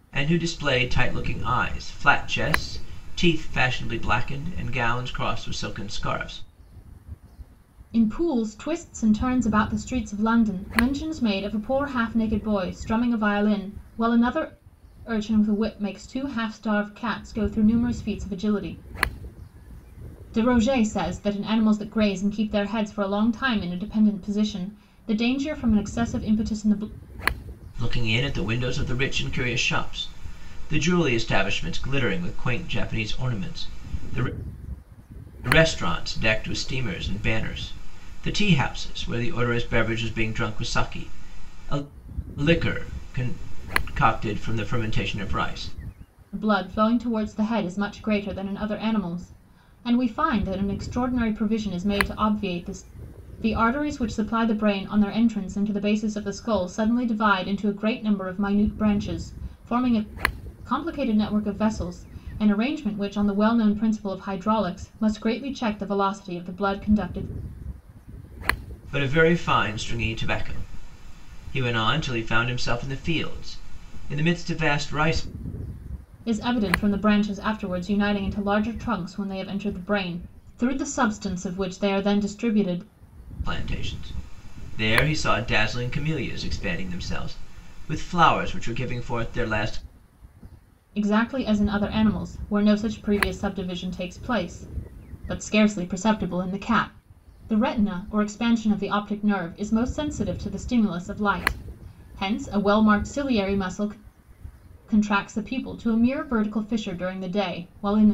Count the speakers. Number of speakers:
2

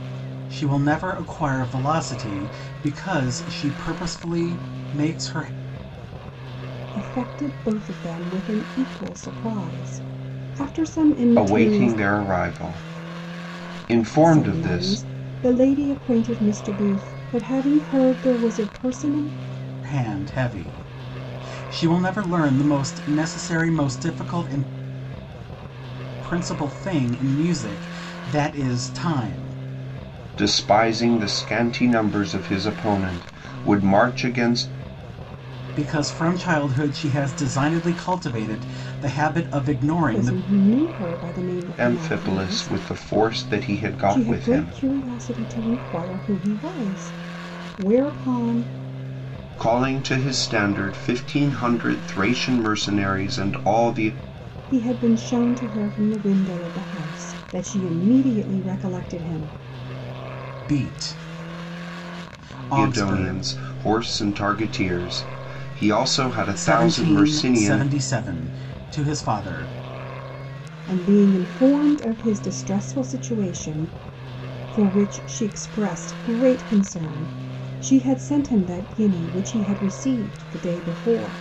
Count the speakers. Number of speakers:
3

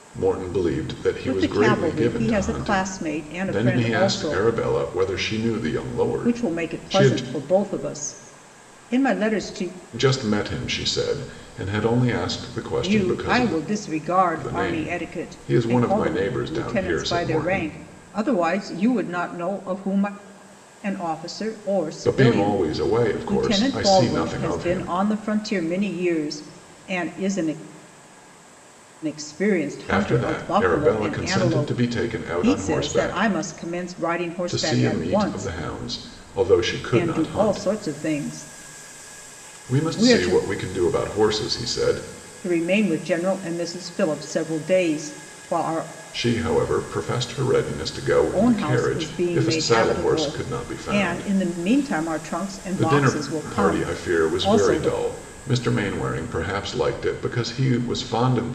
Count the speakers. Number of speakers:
2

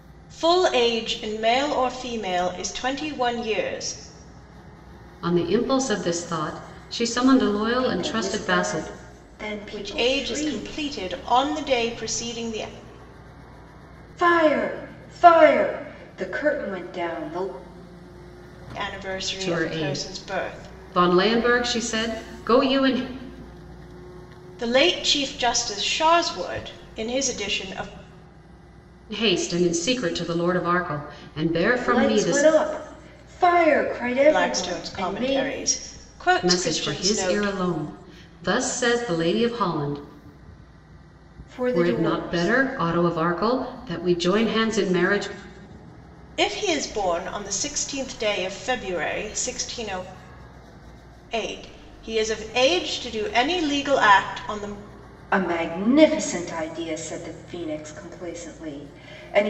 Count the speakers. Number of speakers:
3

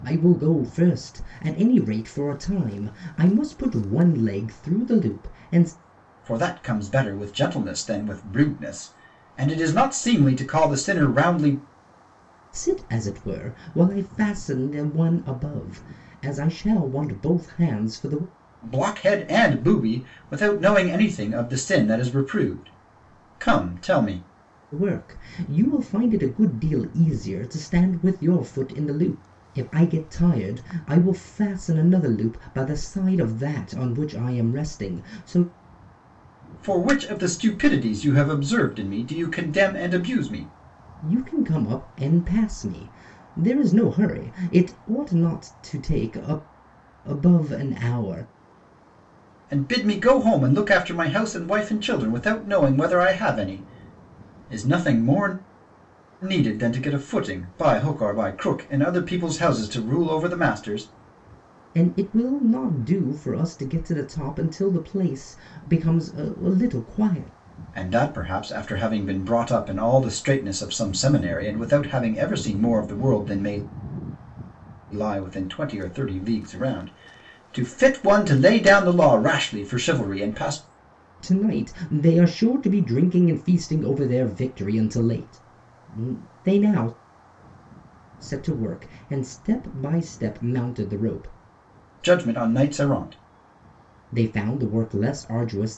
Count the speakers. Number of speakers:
2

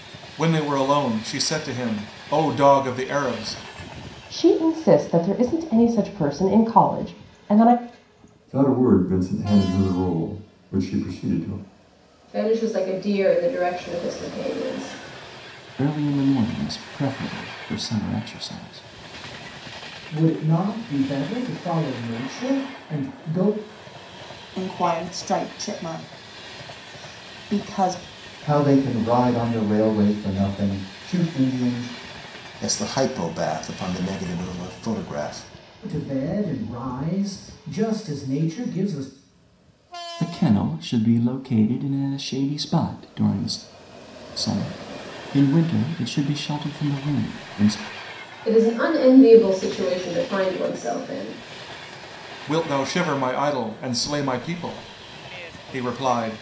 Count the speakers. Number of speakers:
9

